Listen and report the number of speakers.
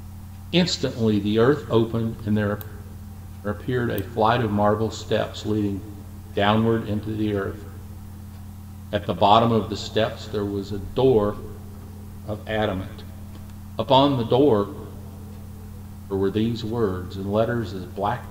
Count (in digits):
1